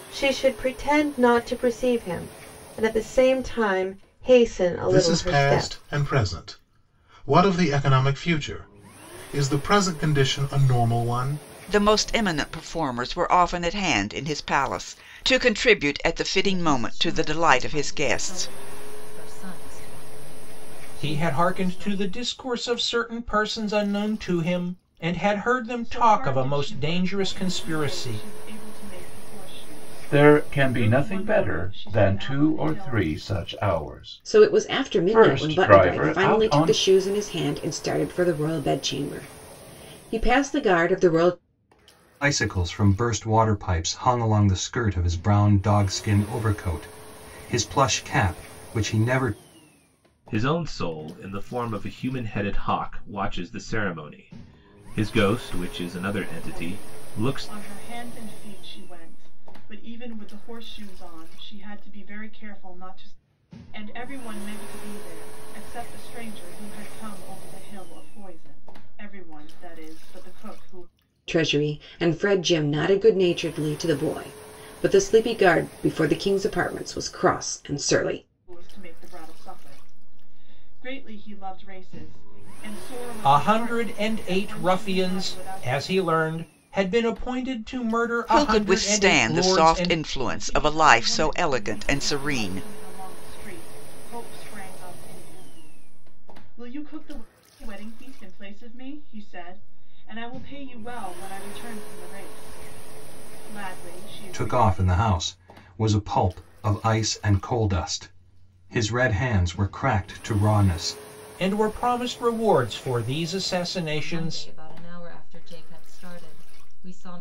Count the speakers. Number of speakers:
ten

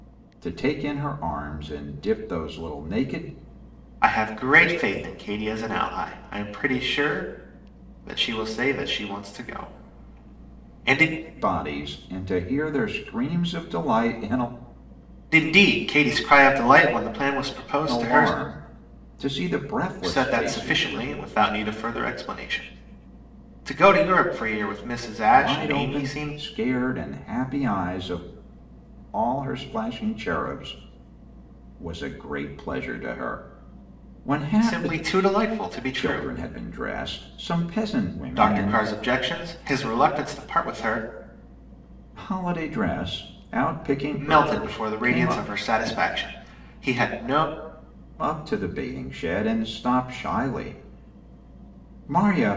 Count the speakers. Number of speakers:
two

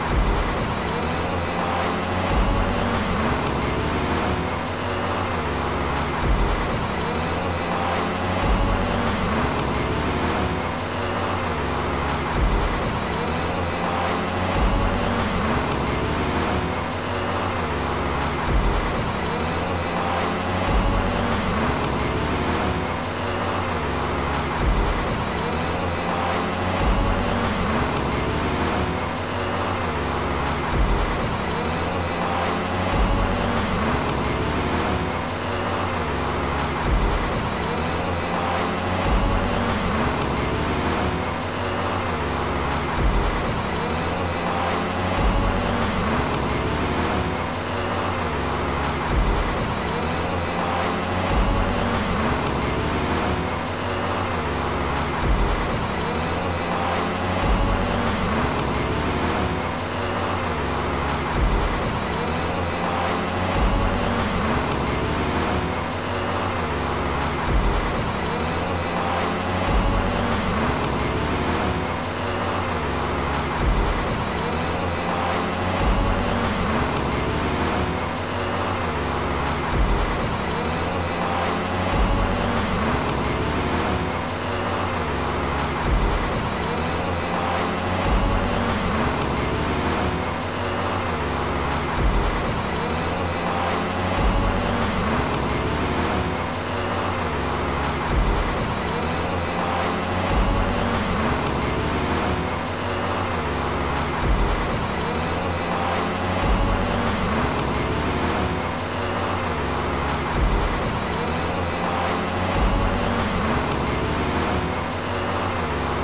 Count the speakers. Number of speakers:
zero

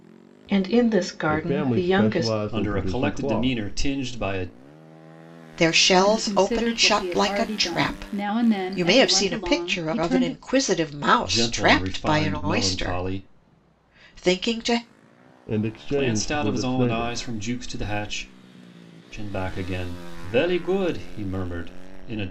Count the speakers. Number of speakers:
five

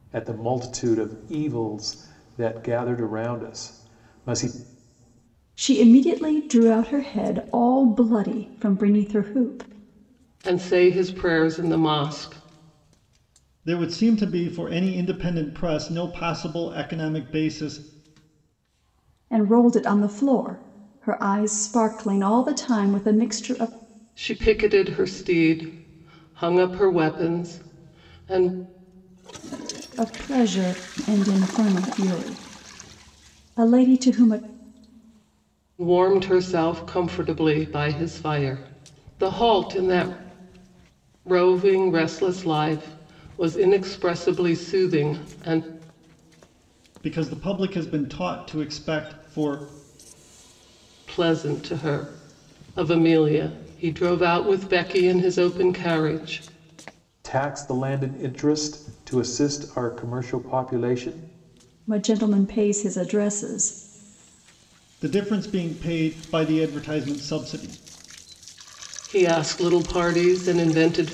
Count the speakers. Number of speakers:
four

